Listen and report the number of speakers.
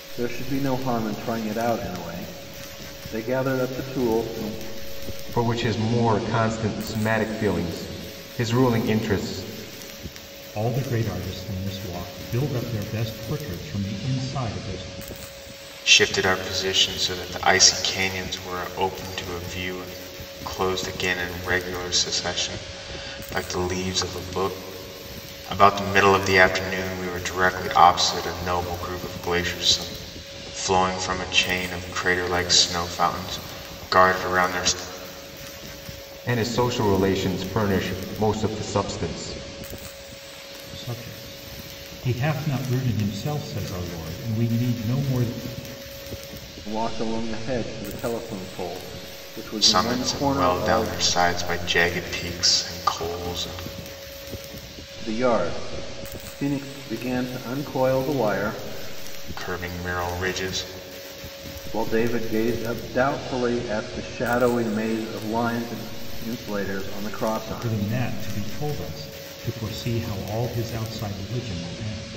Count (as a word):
four